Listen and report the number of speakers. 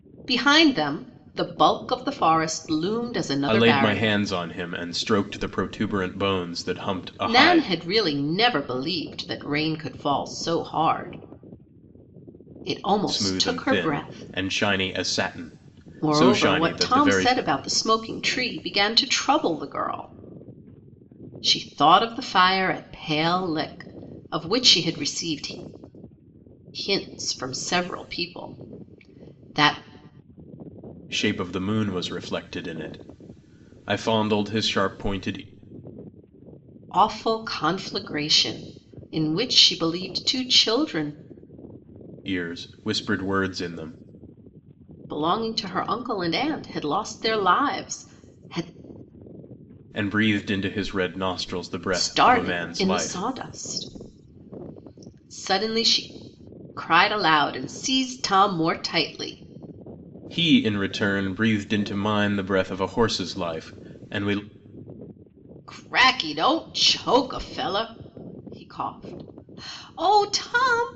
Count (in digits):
2